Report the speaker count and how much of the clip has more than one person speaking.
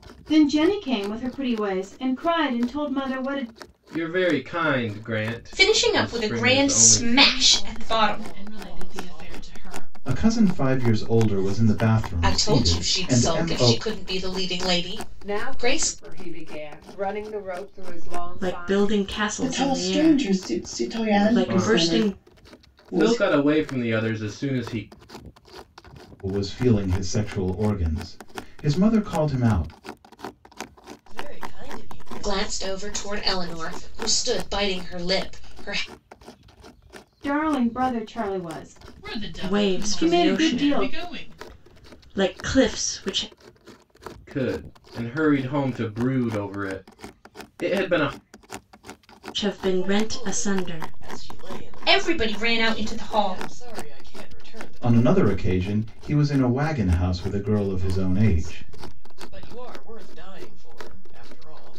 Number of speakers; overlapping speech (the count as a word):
ten, about 36%